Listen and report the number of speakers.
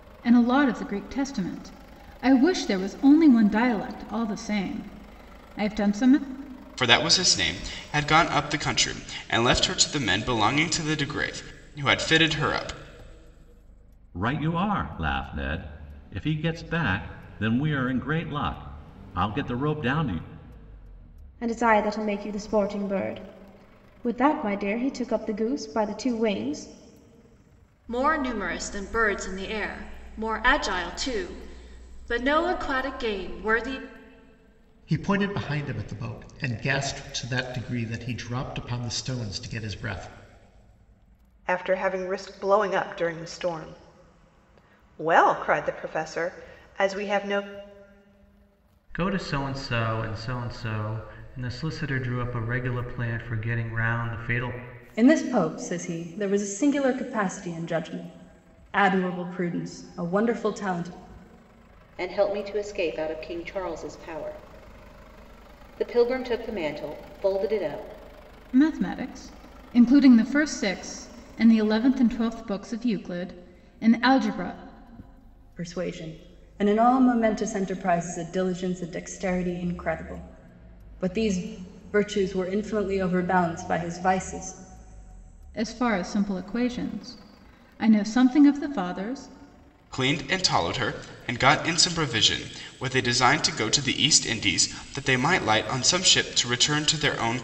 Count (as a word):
ten